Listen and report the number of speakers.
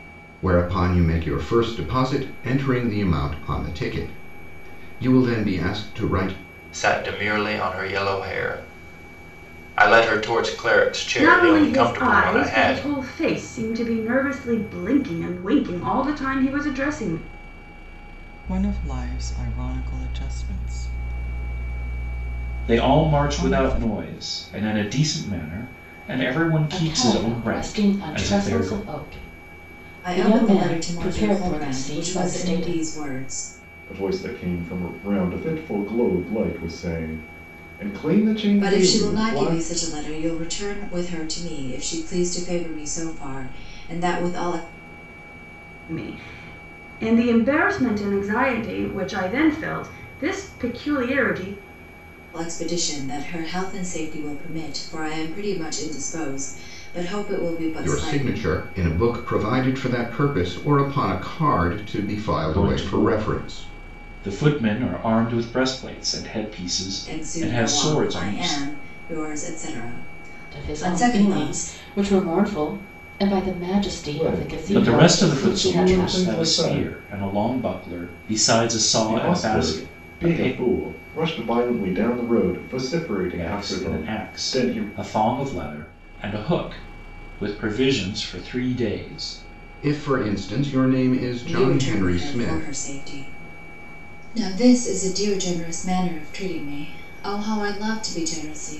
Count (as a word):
eight